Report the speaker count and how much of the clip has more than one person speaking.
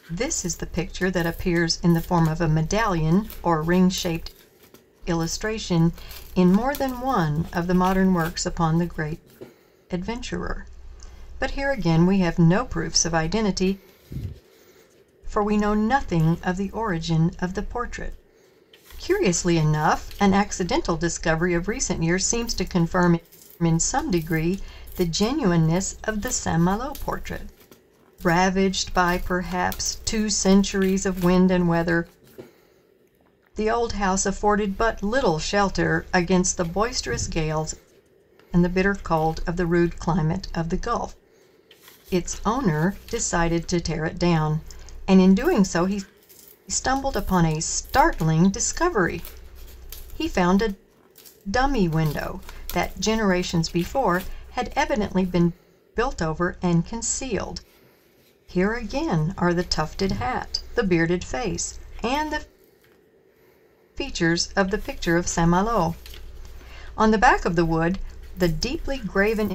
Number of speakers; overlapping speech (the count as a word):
one, no overlap